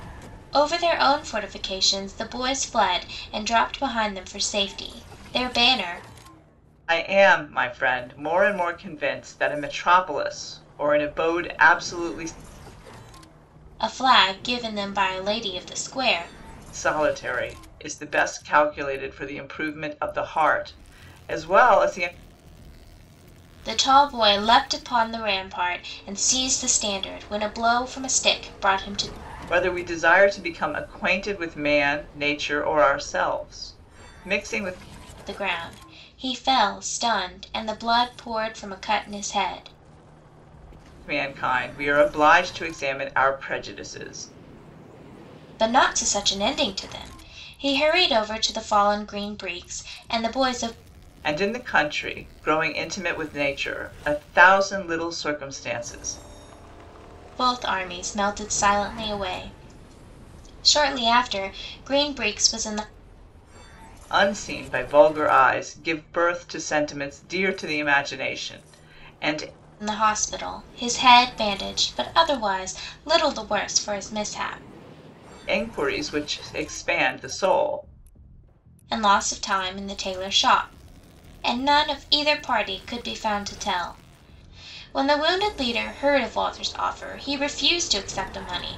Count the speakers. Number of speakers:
2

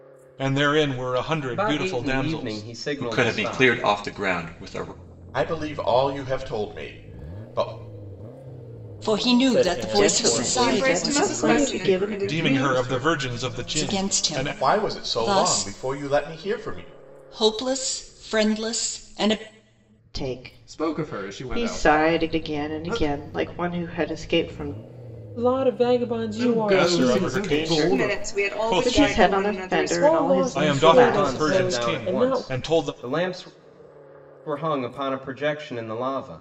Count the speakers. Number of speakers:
9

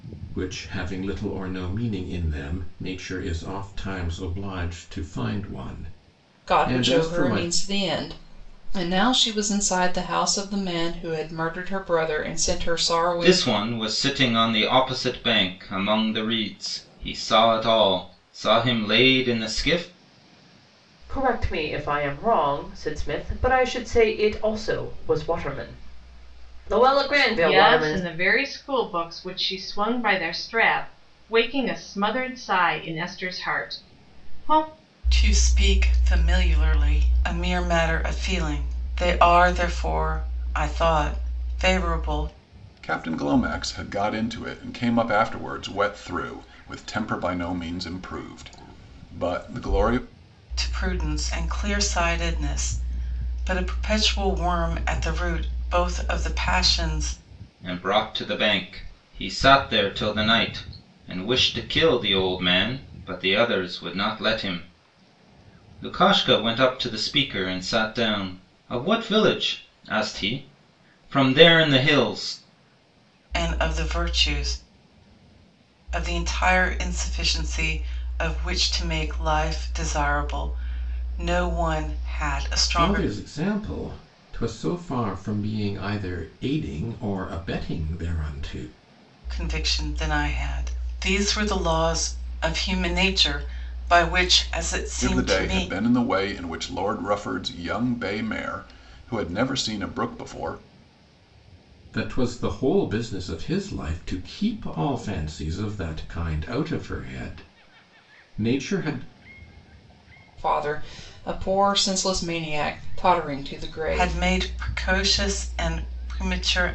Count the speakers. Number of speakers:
7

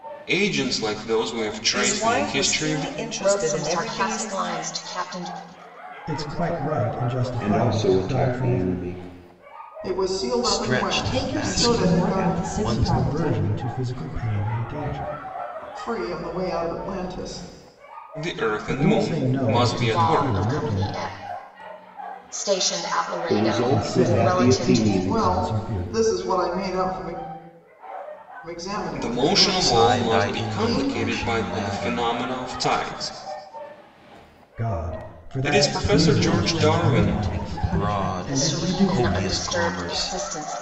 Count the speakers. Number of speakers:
8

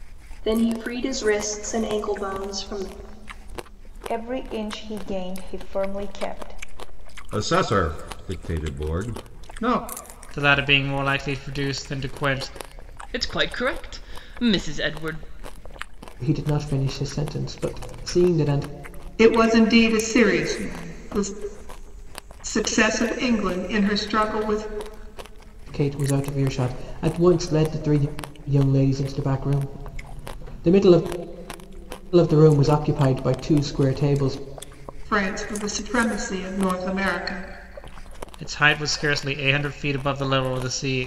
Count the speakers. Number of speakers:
7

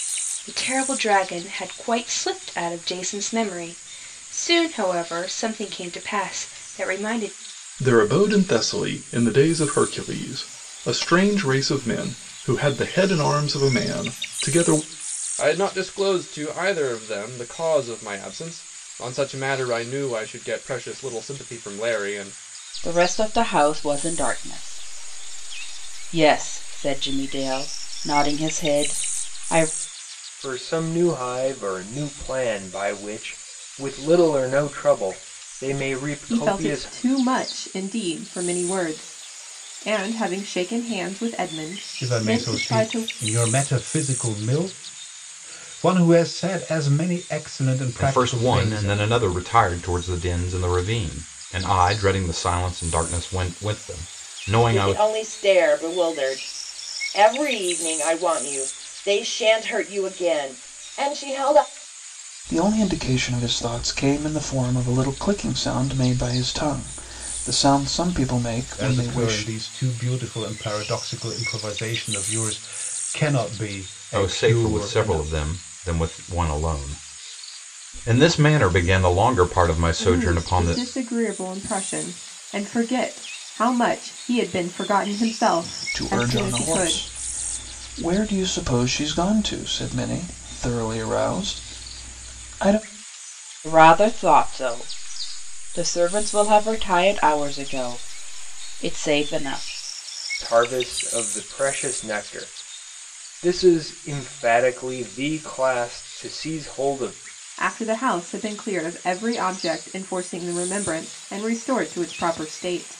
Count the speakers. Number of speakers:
10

